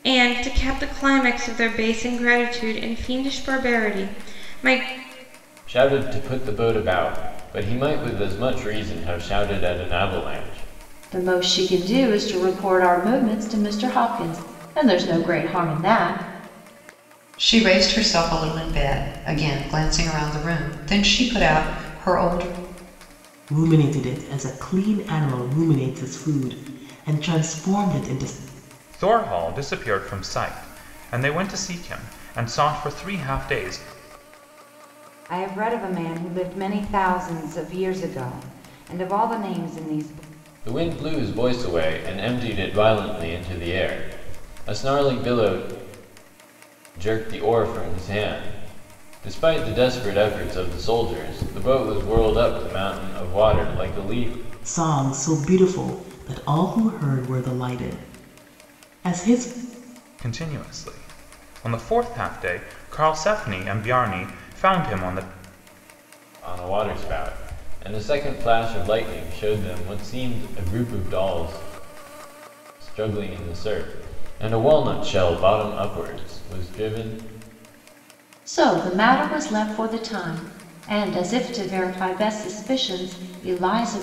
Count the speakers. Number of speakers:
seven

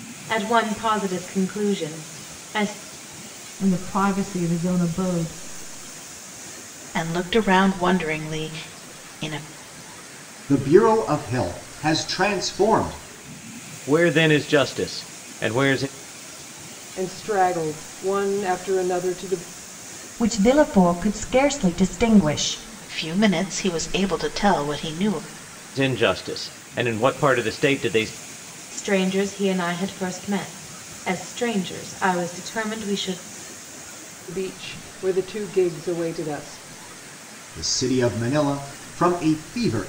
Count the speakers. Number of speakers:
seven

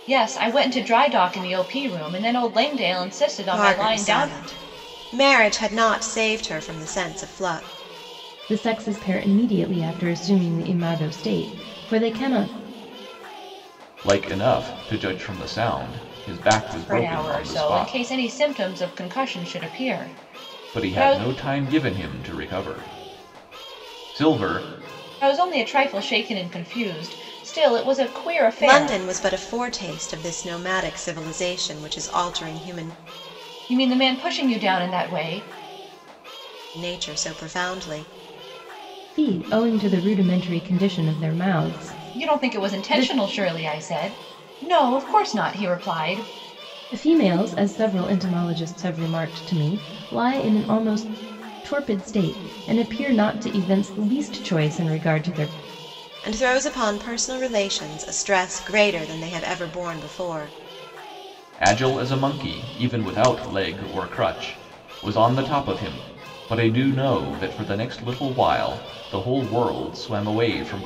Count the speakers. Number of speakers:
four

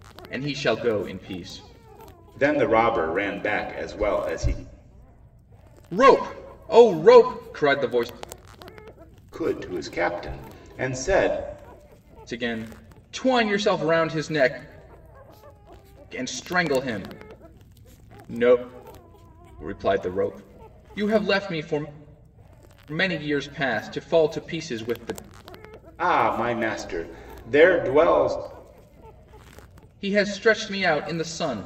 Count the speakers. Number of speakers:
two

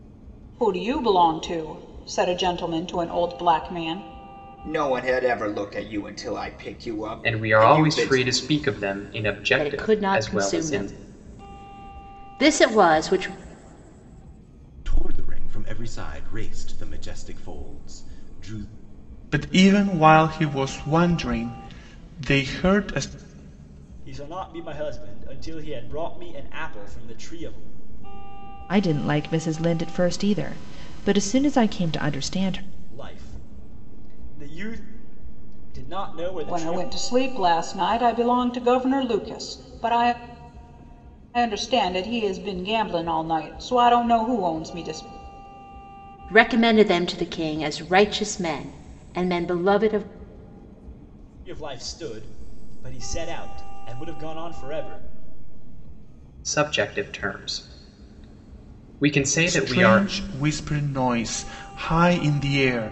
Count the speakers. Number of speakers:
eight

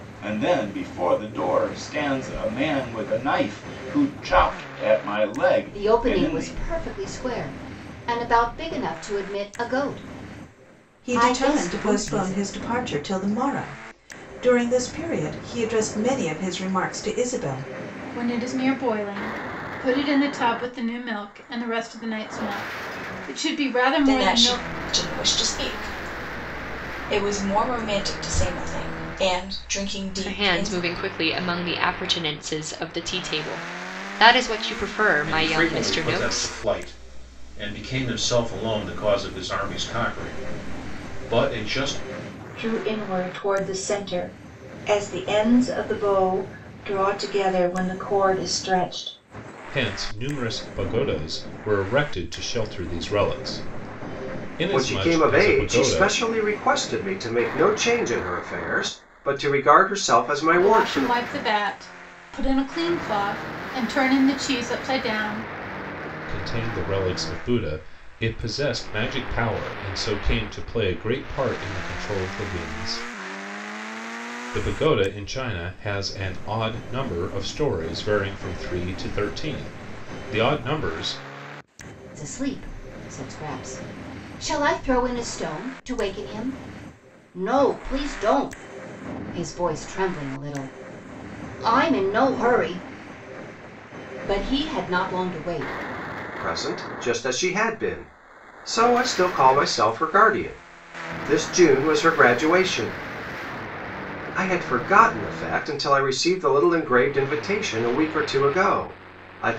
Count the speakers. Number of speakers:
ten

